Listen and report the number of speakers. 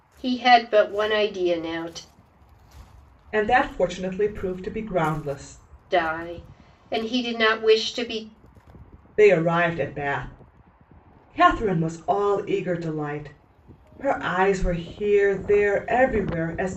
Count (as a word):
two